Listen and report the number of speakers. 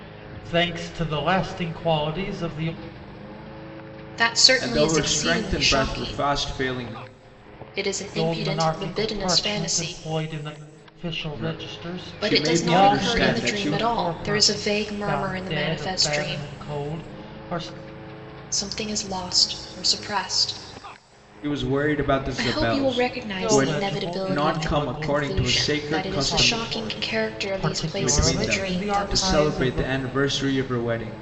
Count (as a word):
three